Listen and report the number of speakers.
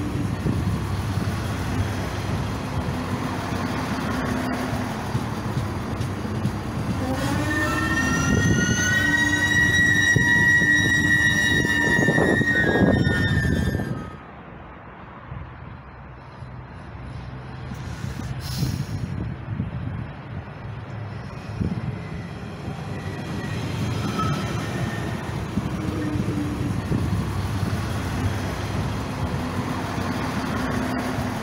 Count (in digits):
0